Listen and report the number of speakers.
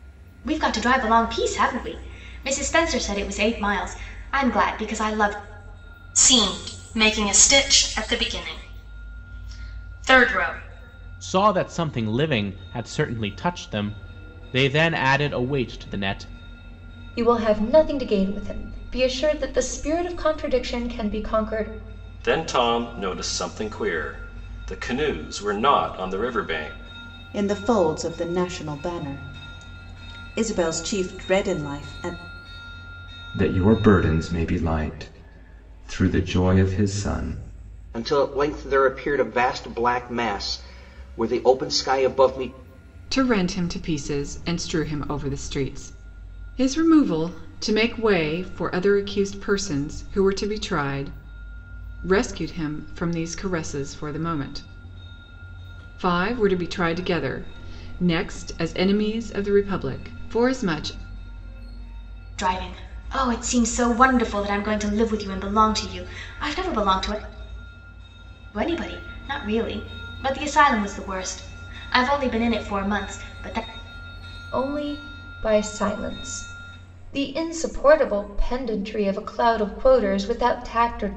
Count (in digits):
9